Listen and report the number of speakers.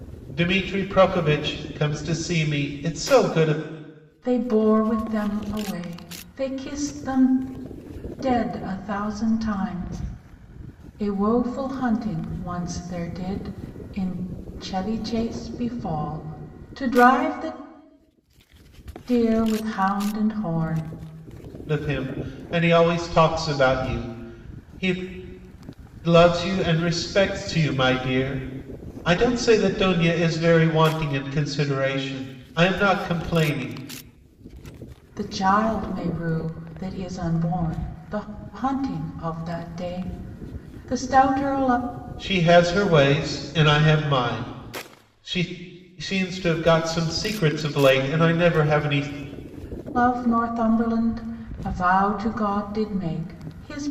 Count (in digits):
2